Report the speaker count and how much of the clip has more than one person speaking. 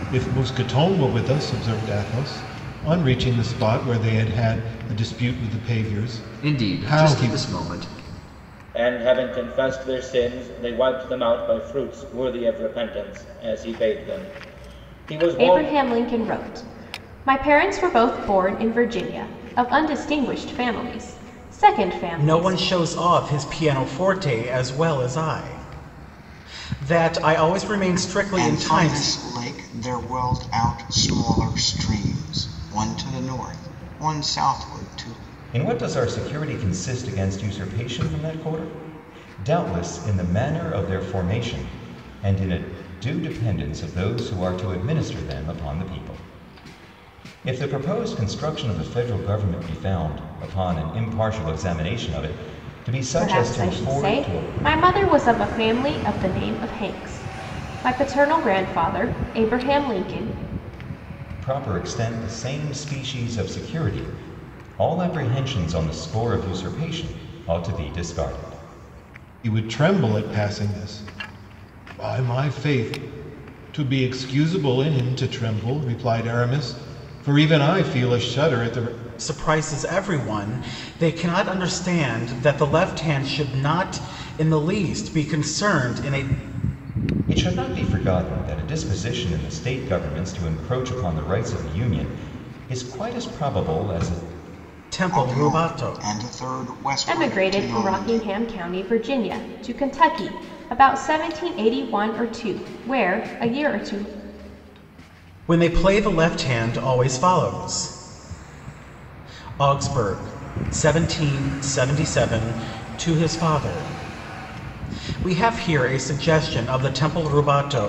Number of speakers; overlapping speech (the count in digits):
7, about 5%